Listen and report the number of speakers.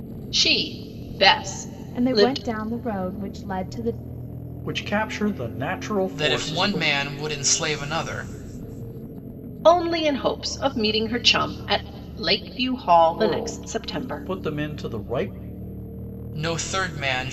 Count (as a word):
four